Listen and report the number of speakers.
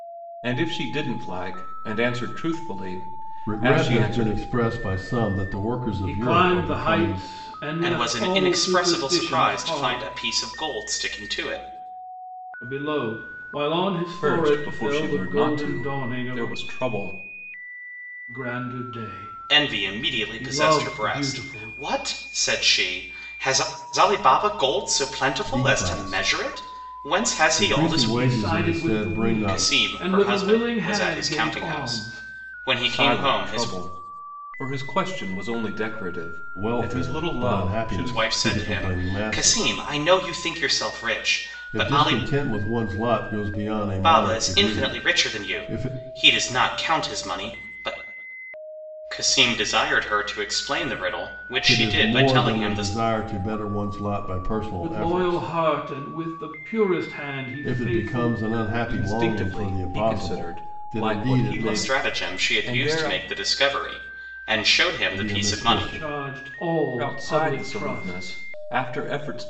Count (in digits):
4